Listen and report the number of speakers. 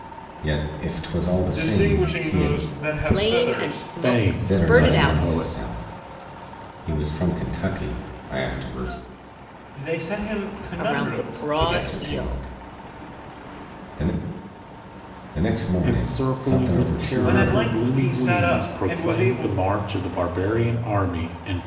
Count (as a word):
four